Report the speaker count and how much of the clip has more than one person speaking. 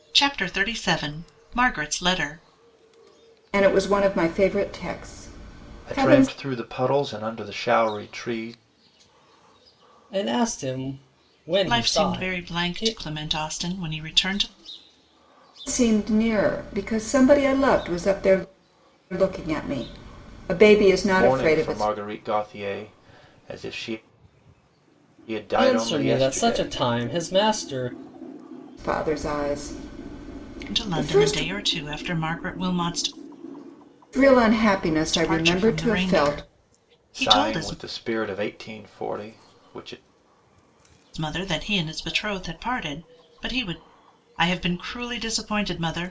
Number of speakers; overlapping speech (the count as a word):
four, about 14%